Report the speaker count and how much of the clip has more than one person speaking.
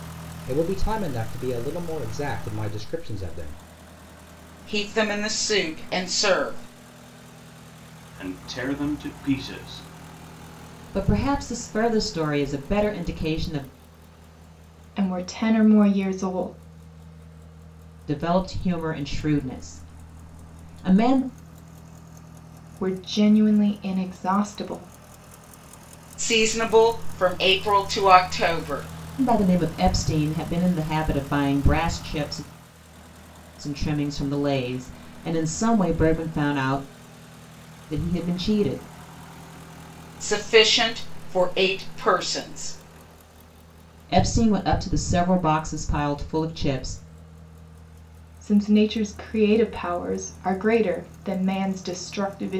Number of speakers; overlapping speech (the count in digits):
5, no overlap